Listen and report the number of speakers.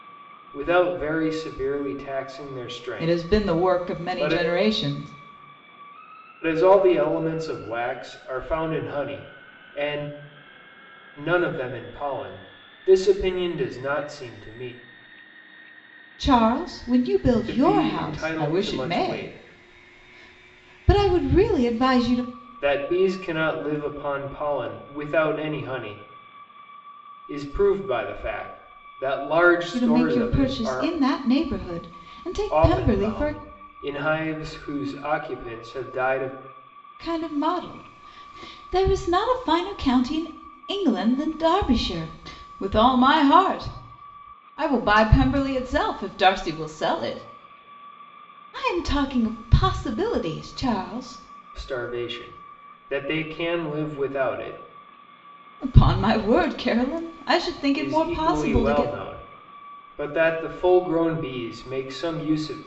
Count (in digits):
2